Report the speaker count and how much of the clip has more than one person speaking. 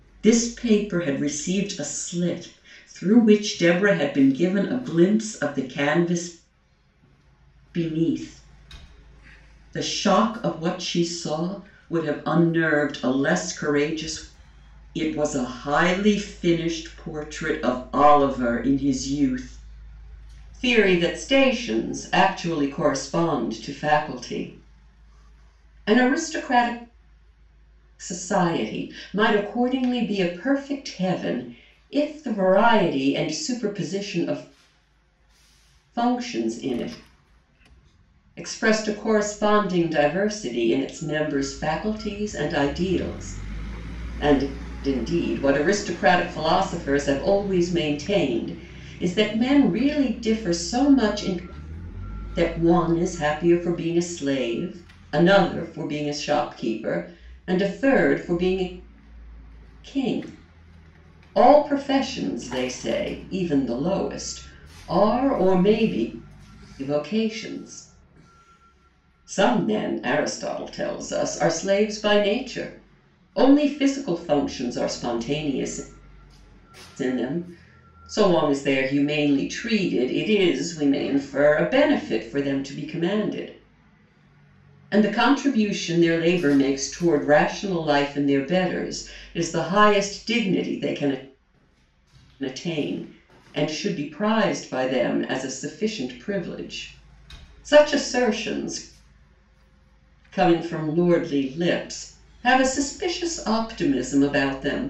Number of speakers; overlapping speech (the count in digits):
1, no overlap